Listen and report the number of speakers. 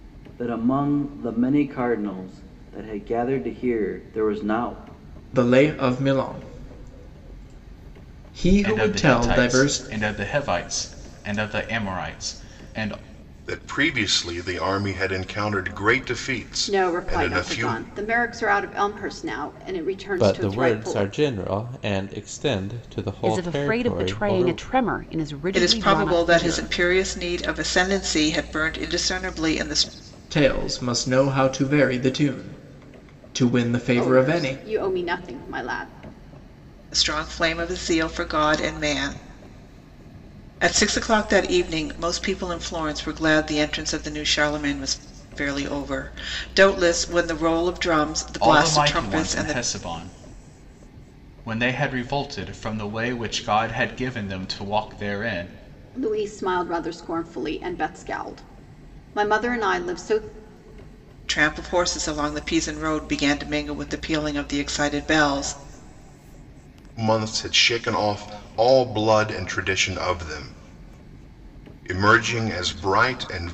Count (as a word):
eight